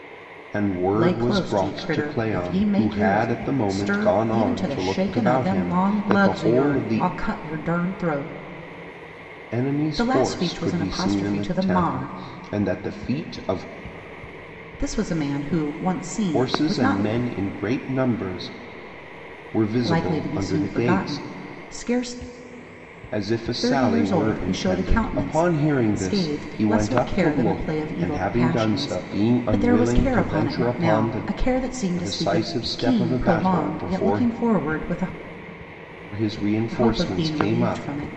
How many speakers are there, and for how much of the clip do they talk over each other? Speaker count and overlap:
two, about 54%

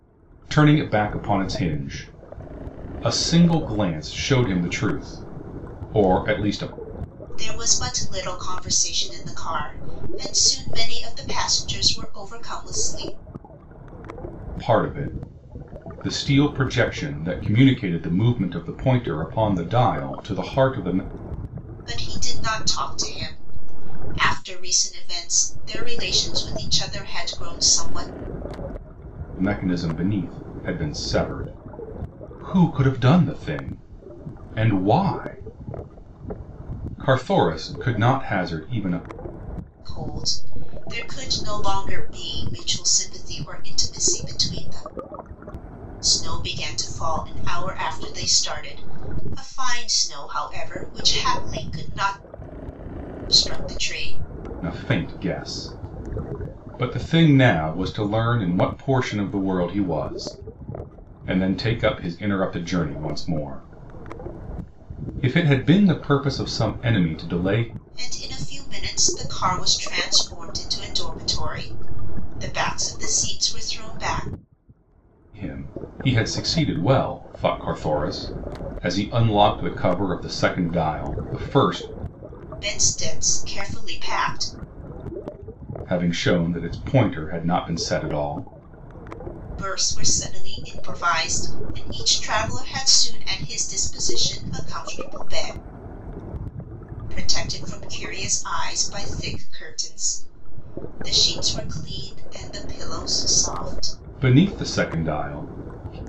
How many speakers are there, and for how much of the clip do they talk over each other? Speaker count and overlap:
two, no overlap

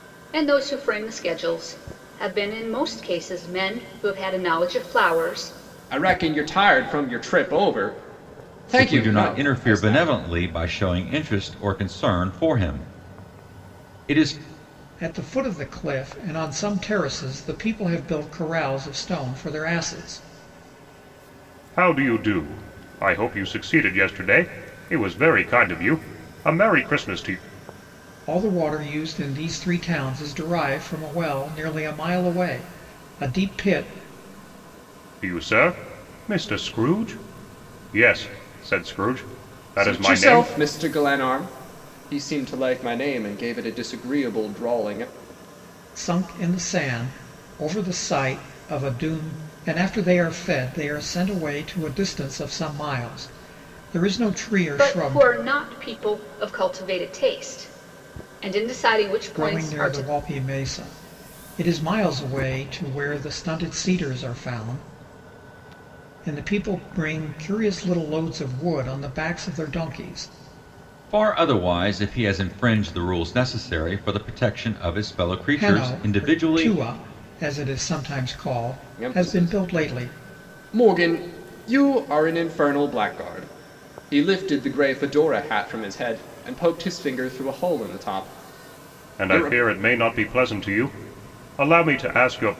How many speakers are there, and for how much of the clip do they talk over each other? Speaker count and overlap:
five, about 7%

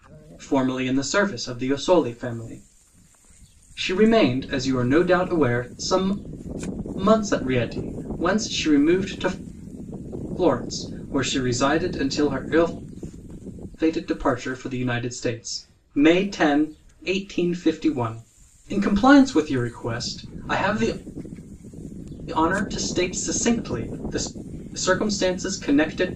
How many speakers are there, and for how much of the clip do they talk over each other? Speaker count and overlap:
one, no overlap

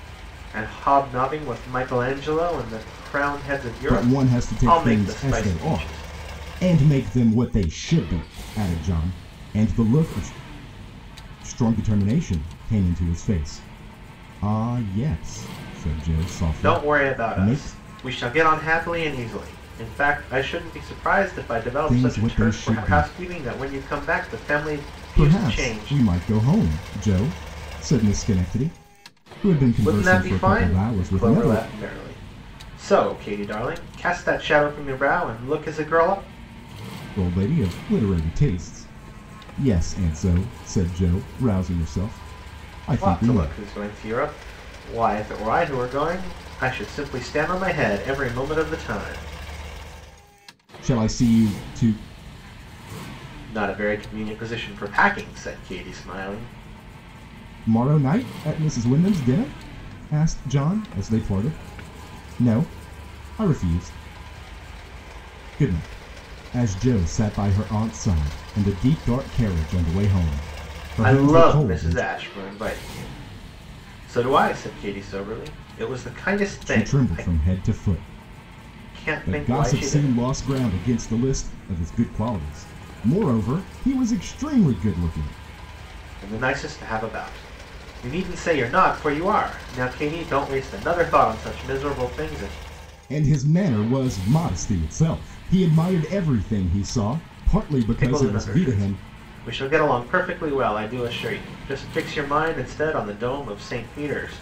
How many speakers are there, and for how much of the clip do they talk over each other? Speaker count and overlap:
two, about 12%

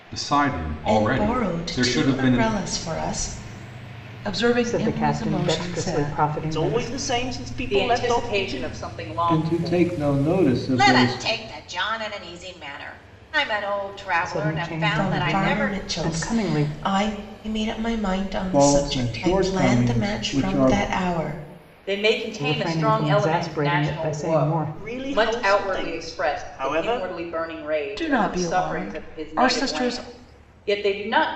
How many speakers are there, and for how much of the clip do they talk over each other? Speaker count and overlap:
eight, about 57%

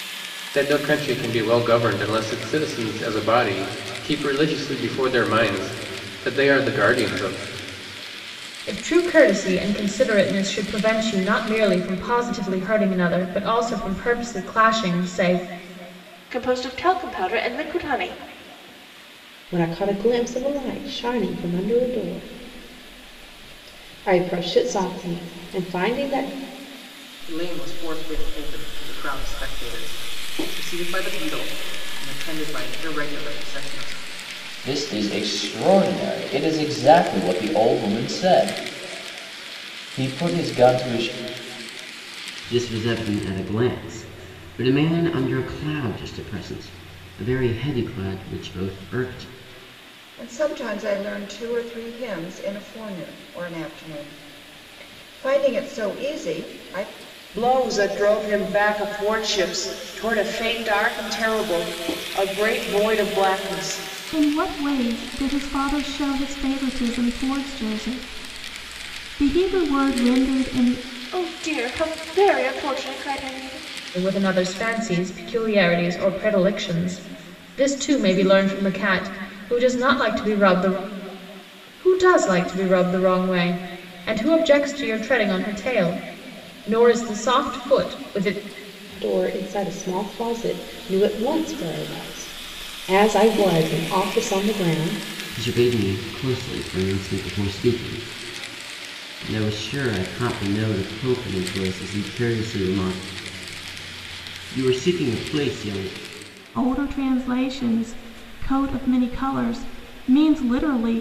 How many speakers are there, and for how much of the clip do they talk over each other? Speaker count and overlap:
ten, no overlap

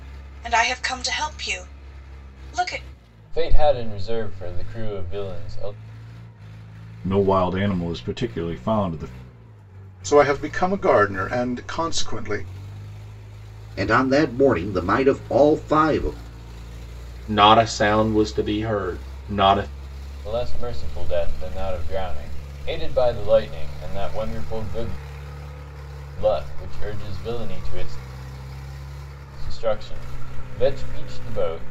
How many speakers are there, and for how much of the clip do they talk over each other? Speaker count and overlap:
six, no overlap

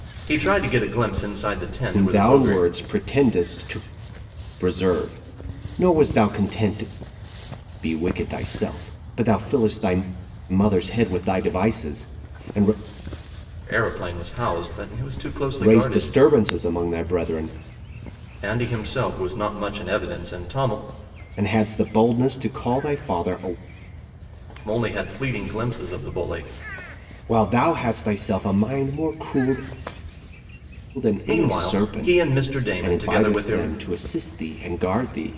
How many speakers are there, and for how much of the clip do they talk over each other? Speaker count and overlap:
two, about 9%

